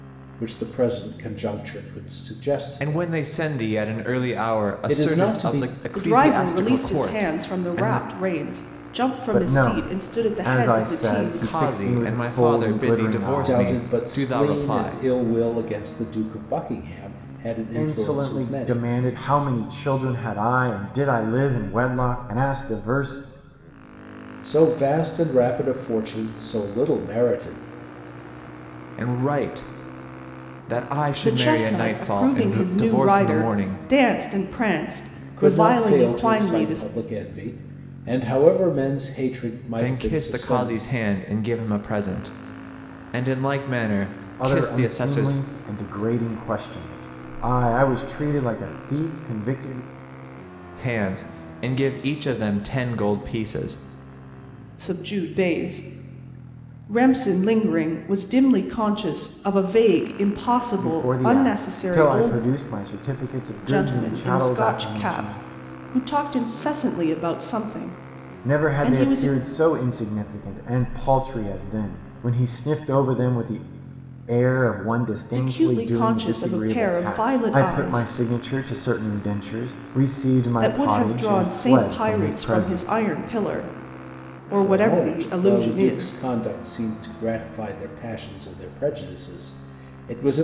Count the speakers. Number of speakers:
4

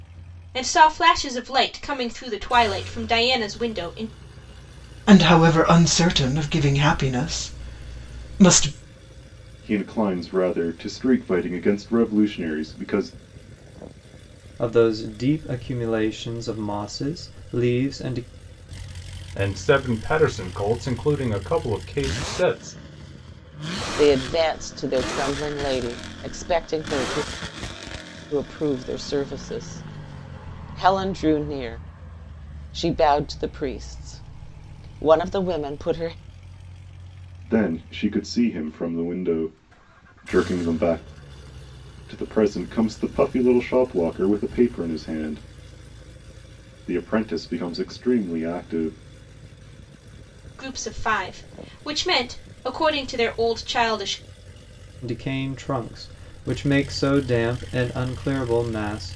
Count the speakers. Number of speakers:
6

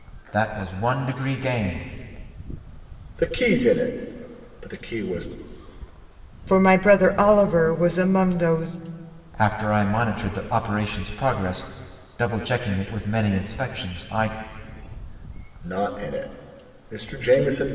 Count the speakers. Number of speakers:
3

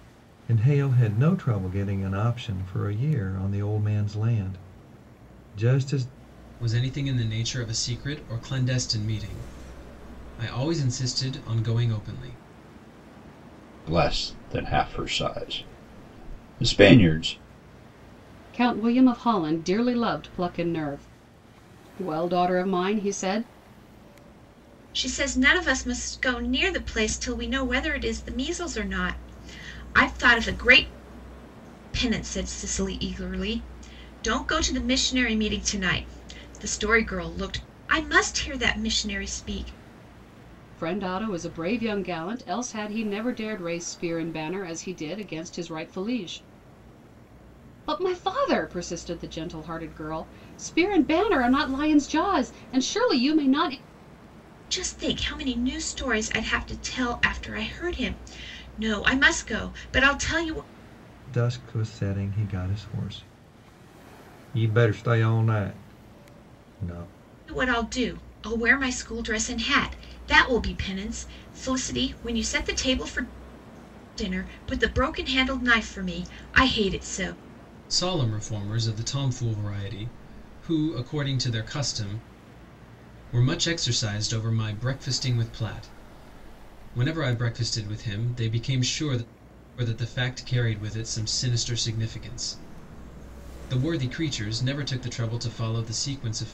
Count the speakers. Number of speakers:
5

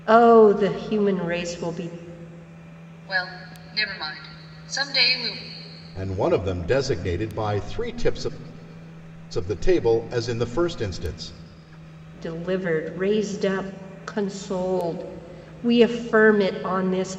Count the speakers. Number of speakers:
3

